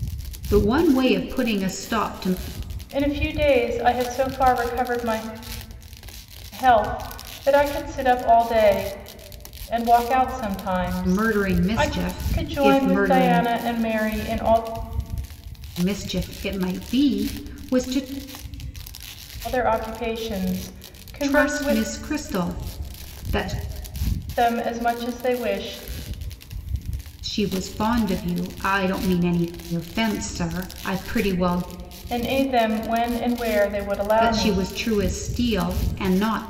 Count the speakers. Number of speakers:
2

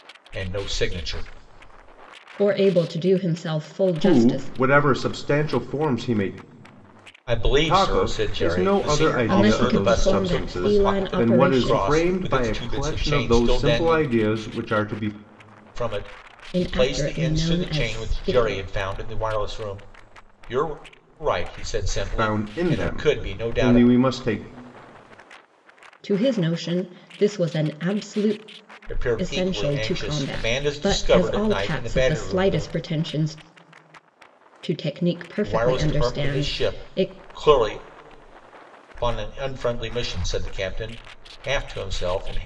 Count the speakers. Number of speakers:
3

